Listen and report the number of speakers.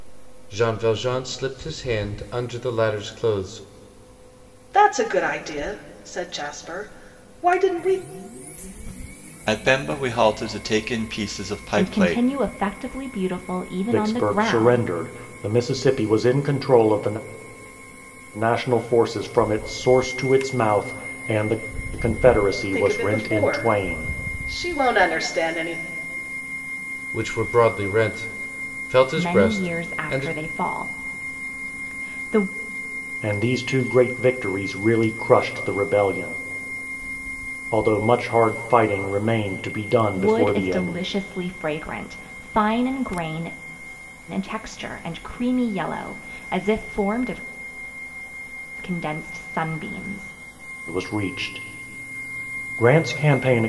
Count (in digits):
5